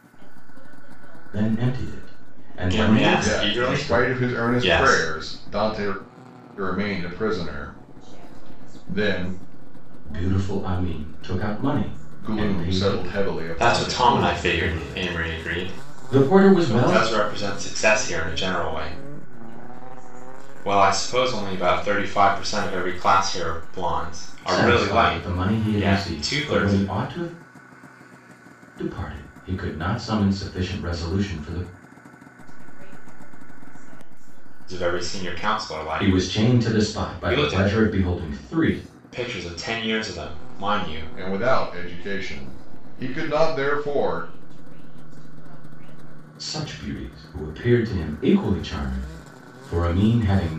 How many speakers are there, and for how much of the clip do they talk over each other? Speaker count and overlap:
four, about 53%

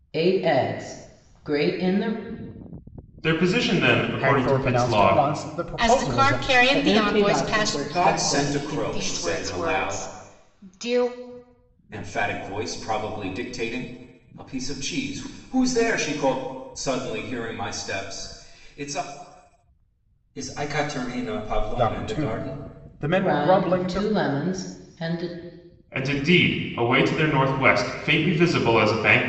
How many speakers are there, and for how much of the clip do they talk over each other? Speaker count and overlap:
seven, about 24%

